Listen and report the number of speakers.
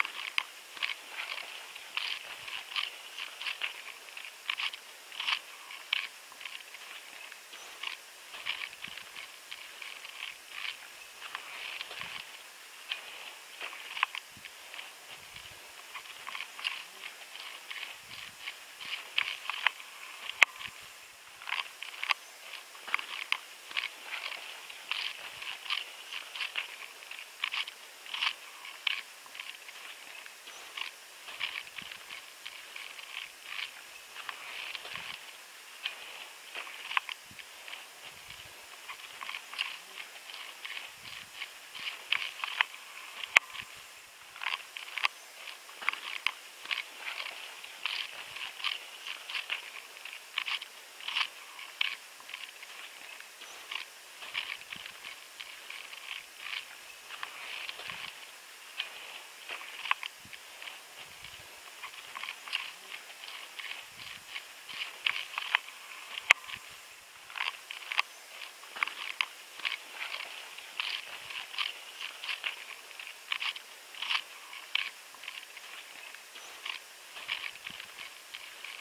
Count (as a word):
zero